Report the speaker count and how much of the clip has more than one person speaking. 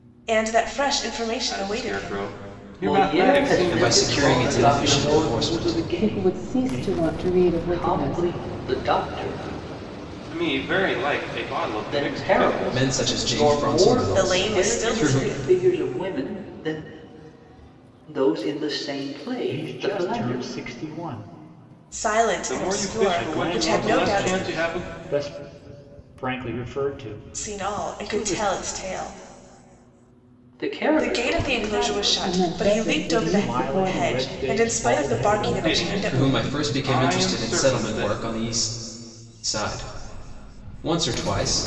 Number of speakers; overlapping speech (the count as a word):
six, about 51%